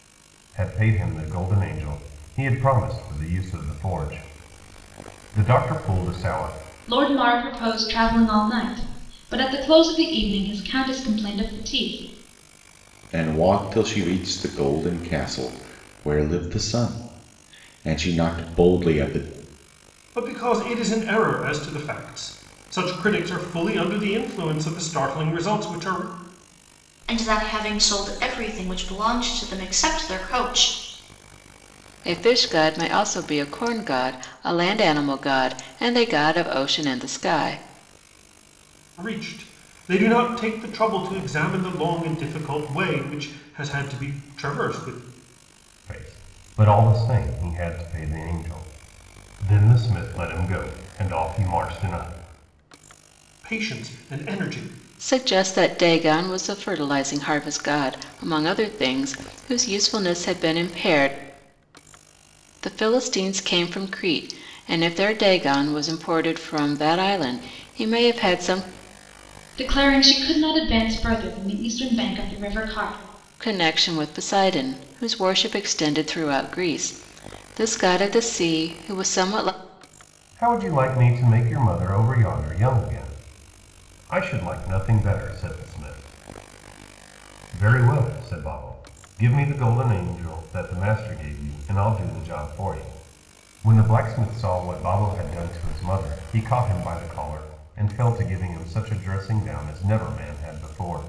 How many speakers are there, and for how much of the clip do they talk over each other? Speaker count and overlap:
six, no overlap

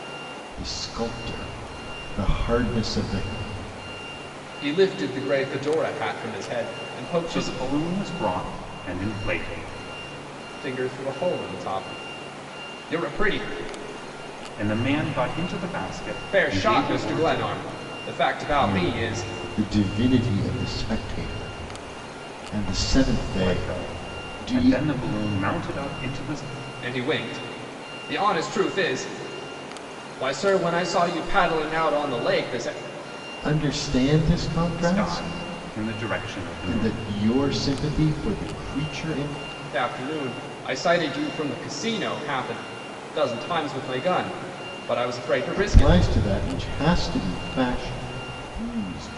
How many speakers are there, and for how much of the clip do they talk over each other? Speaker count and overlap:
three, about 11%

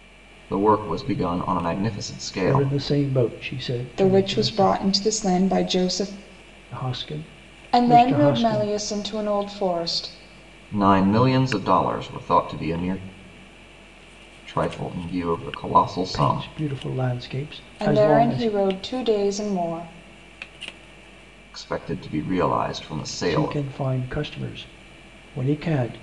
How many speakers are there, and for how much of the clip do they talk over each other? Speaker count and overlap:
three, about 15%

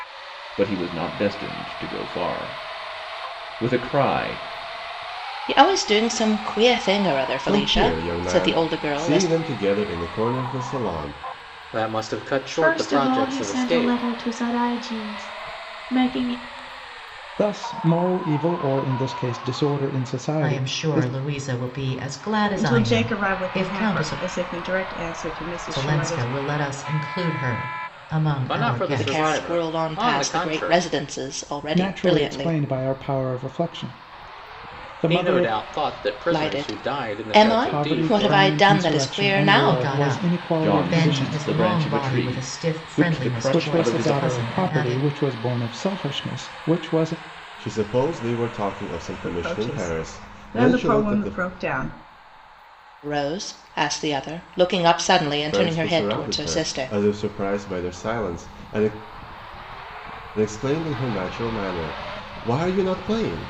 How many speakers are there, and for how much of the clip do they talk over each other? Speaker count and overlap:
eight, about 36%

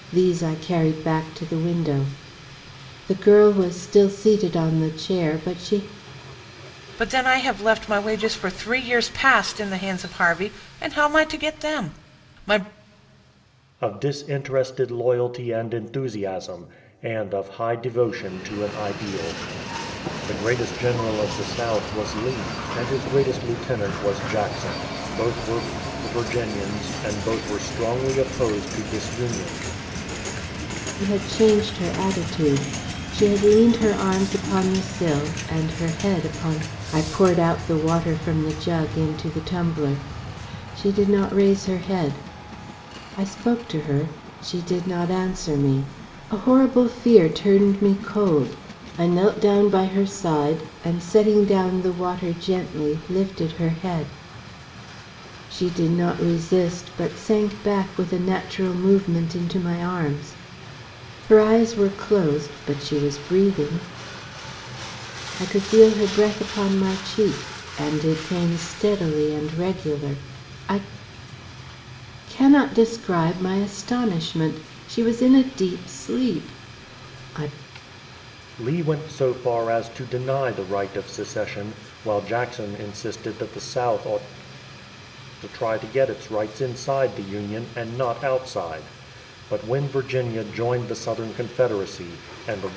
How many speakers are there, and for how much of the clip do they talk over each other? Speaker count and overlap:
three, no overlap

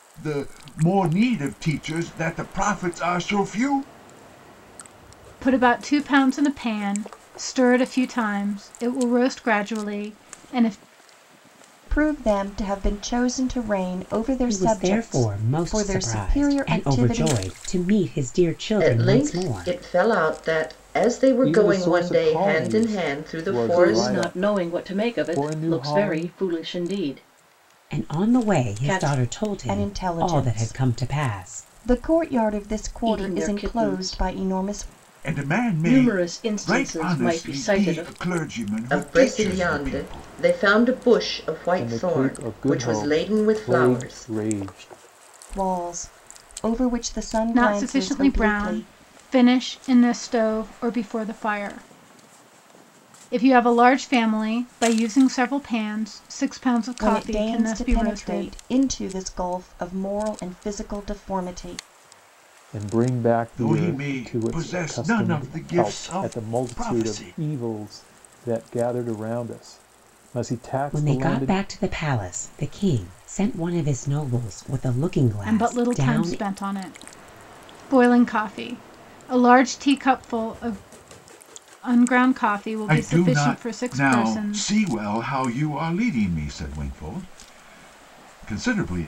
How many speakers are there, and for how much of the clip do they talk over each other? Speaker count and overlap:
seven, about 36%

